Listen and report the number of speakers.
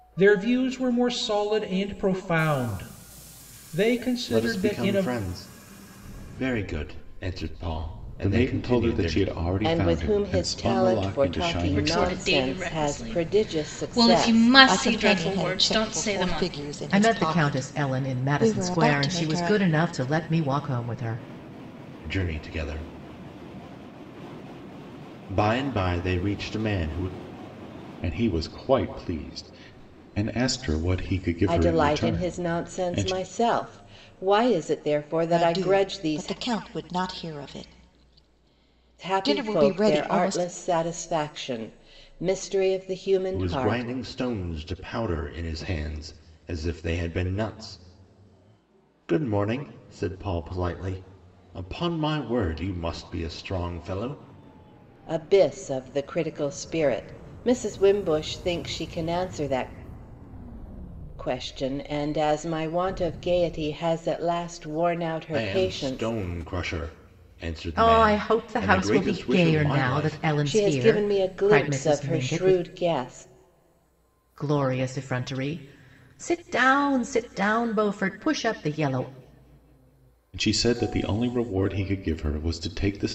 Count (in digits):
7